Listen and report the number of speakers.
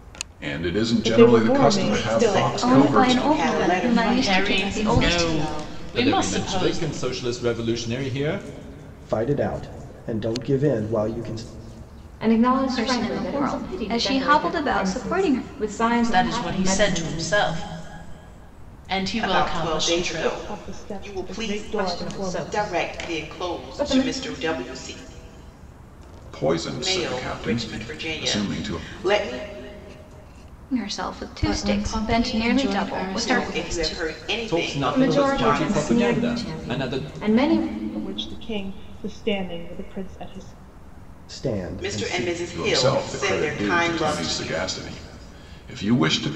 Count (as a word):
nine